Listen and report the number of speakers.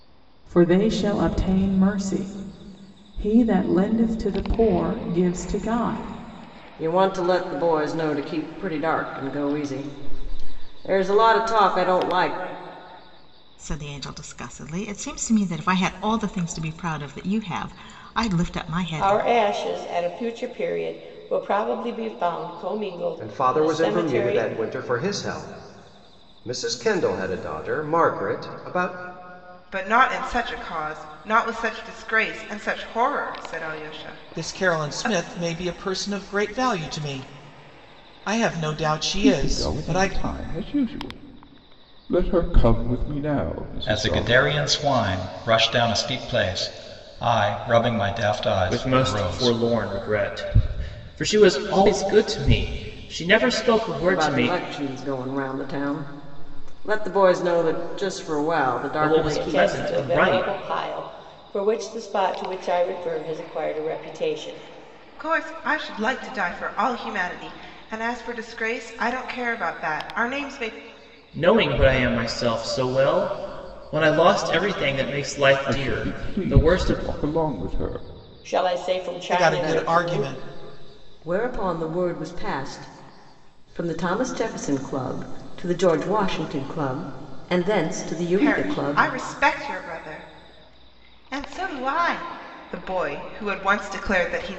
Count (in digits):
10